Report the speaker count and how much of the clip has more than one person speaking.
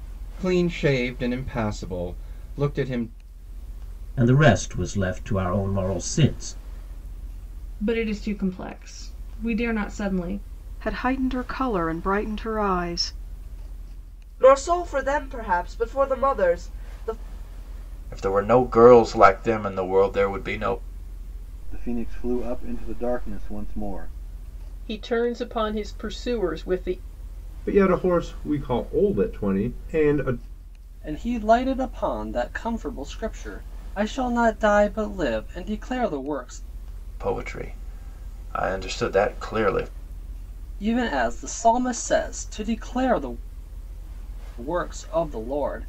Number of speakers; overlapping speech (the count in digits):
10, no overlap